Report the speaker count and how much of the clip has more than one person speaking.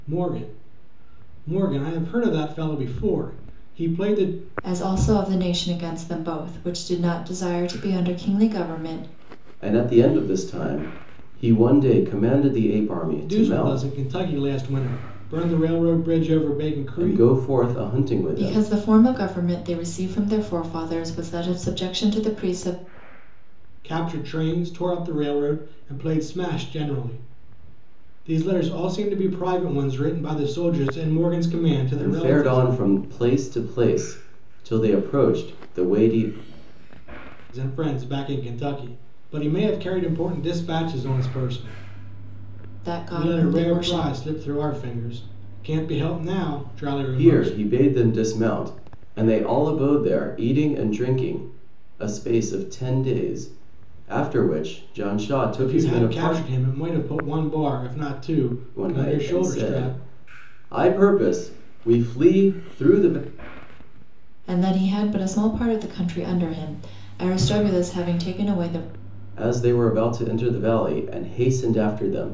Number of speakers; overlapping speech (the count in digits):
3, about 8%